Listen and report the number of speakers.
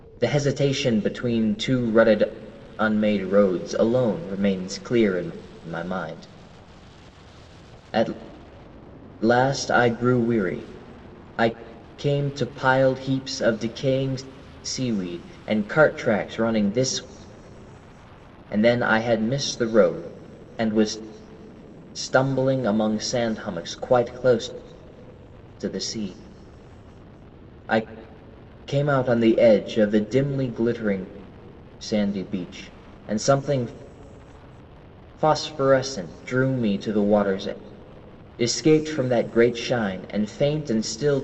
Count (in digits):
1